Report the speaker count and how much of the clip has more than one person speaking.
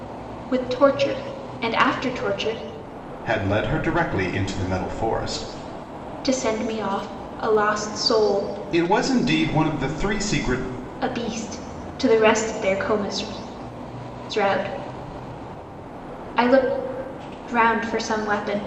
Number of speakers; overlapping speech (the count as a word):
two, no overlap